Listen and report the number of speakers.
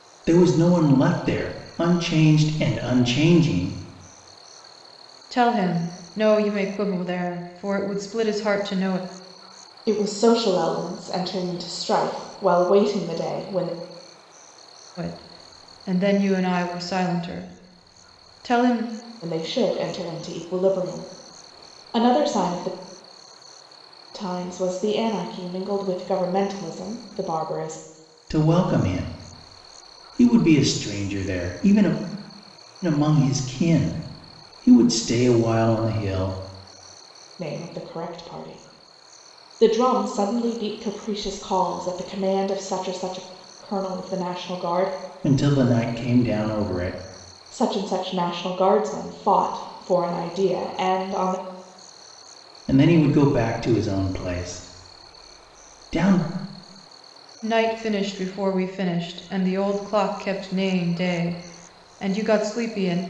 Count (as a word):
three